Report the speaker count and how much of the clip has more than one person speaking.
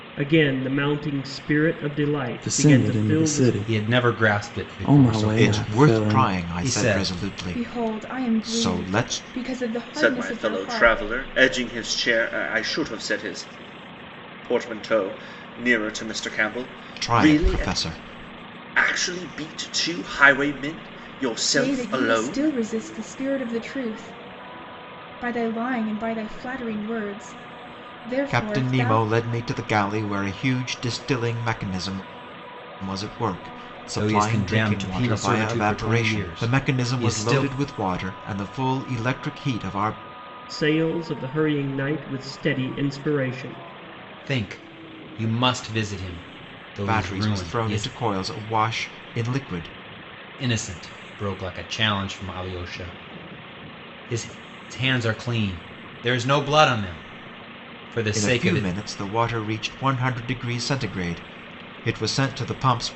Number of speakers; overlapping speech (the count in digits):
6, about 25%